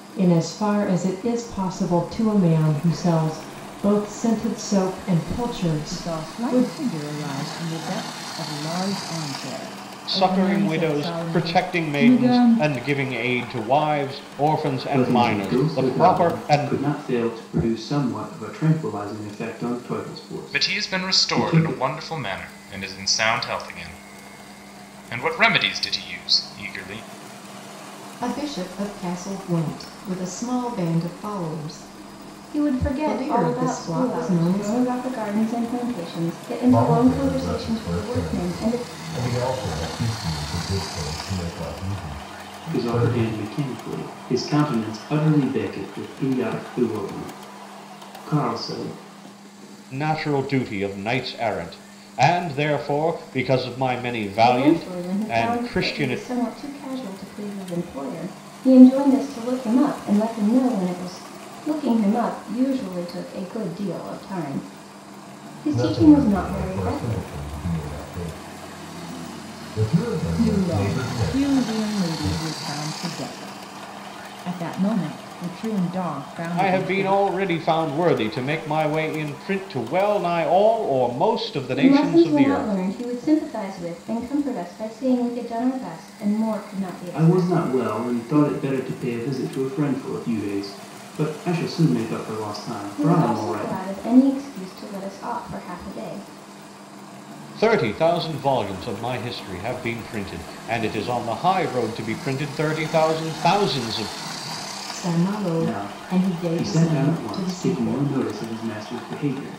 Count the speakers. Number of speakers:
8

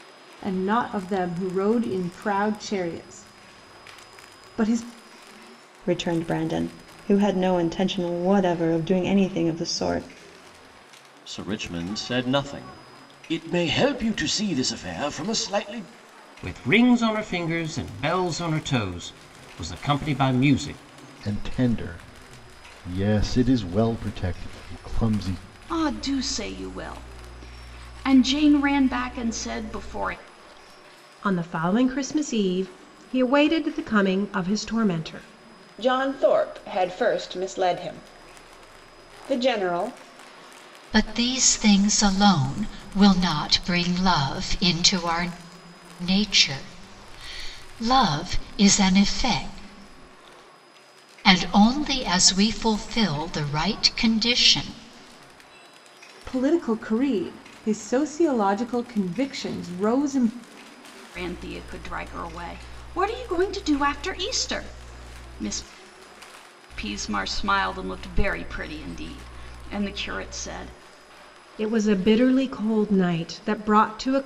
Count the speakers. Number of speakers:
9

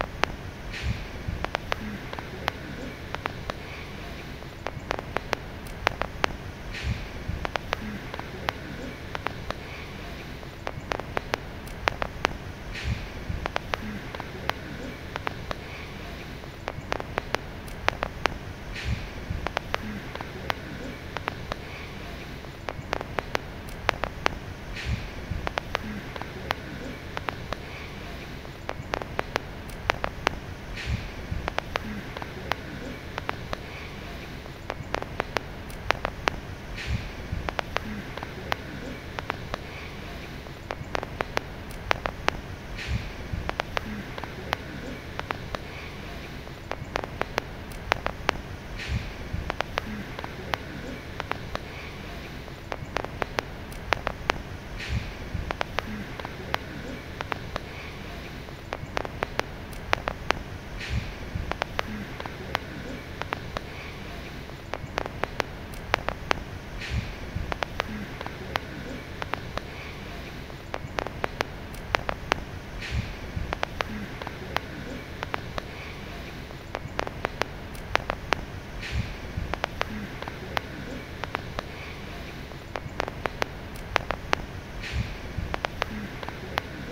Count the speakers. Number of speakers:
0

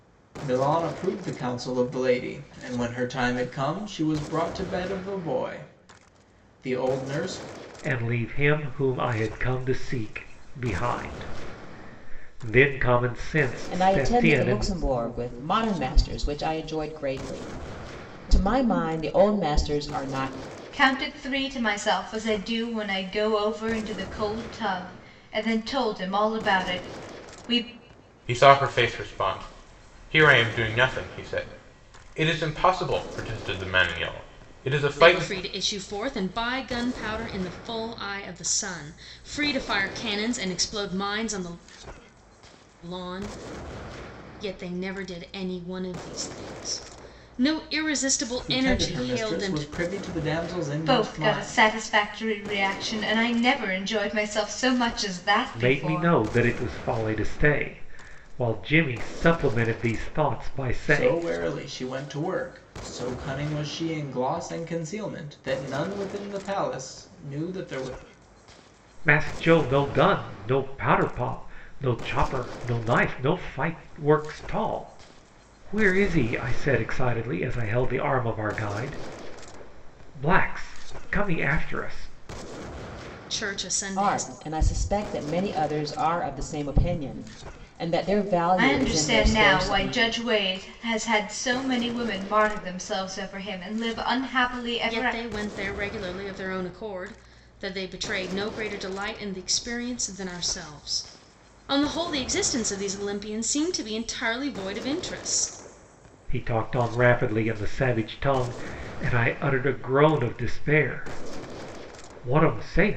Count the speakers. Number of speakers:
6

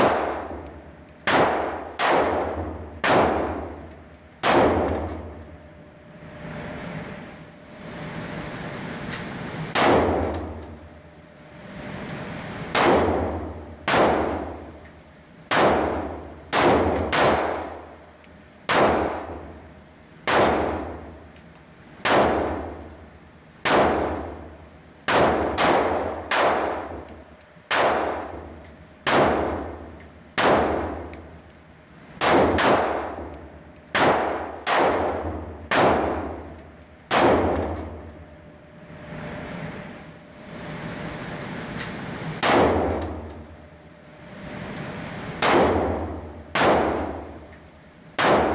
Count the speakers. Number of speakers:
0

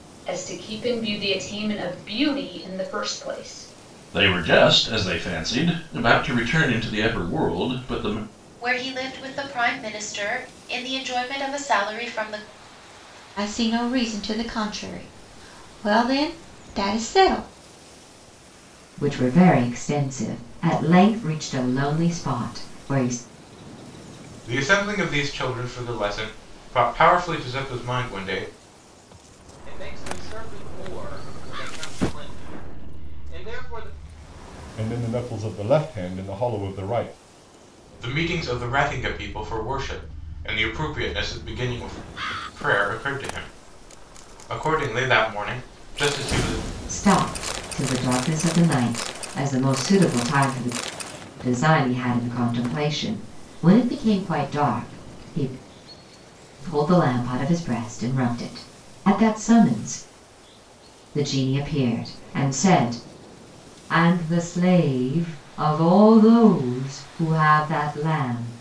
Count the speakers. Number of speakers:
8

